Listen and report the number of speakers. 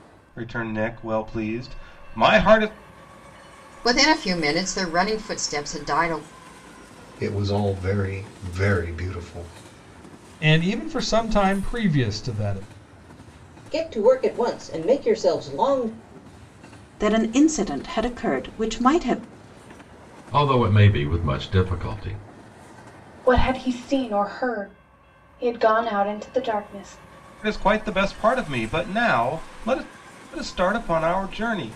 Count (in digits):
8